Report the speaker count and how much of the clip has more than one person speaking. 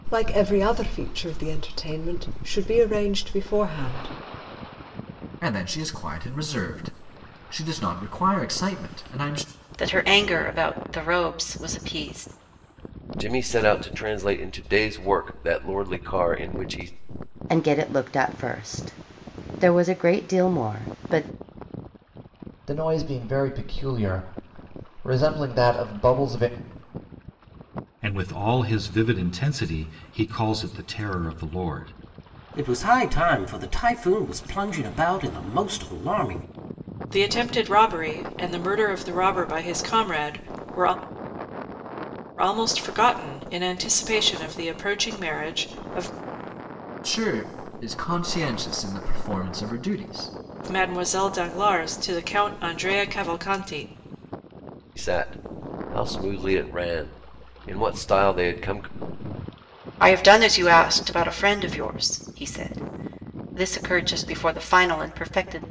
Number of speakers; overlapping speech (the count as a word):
nine, no overlap